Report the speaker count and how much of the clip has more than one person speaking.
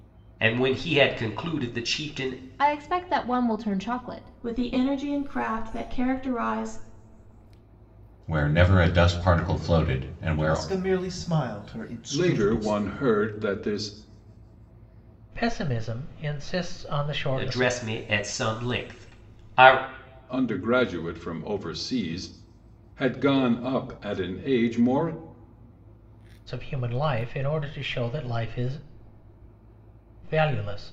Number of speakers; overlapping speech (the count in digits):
7, about 6%